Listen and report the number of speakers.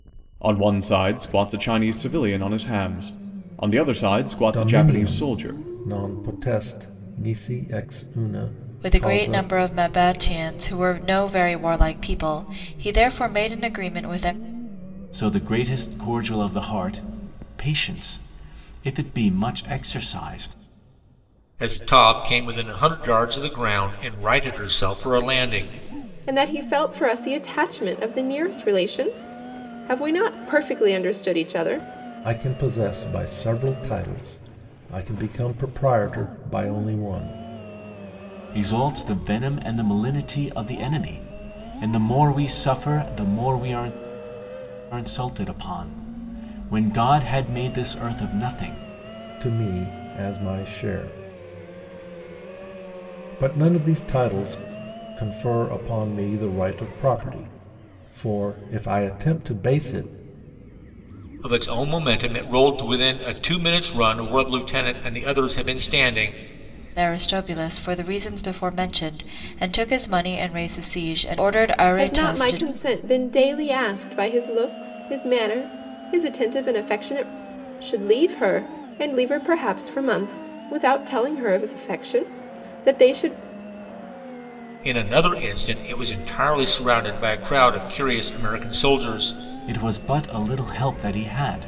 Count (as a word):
six